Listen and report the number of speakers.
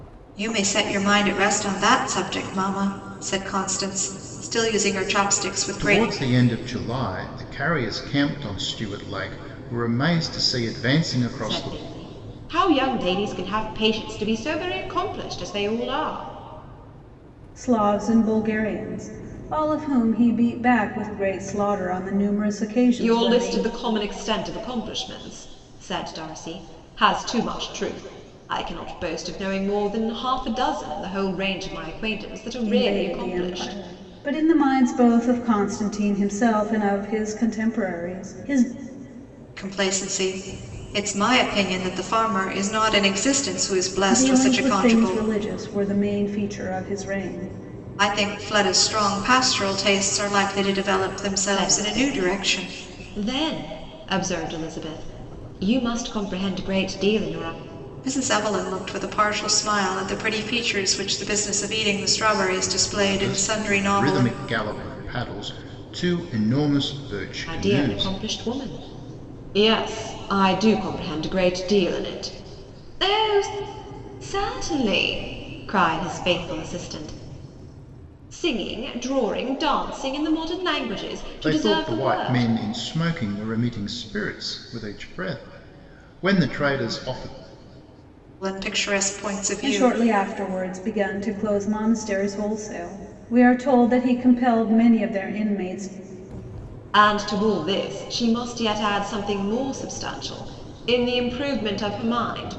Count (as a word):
four